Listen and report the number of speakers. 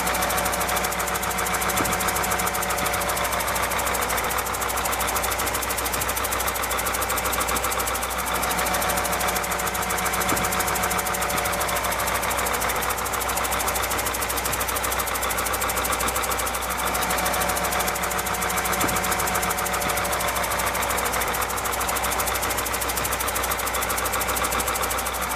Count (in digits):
0